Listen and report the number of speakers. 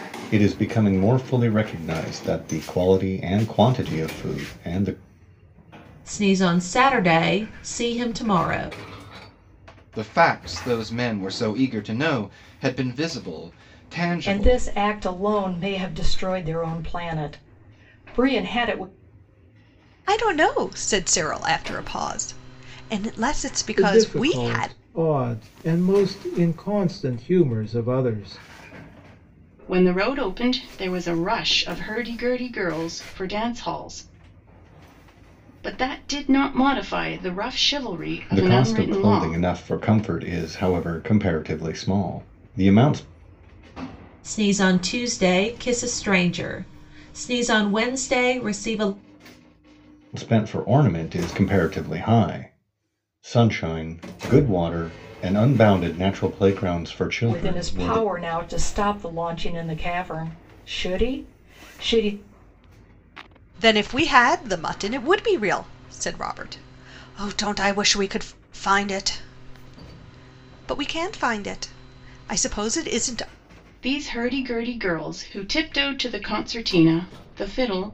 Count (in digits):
7